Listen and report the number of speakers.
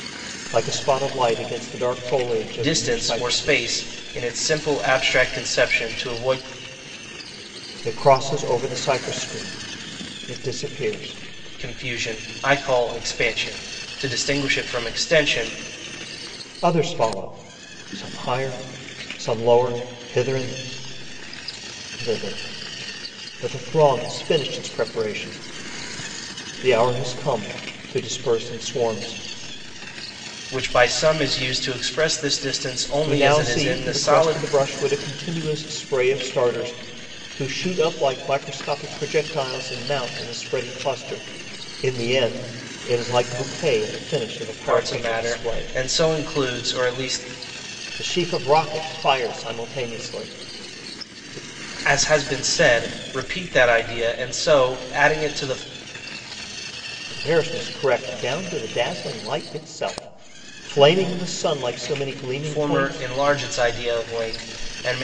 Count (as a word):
two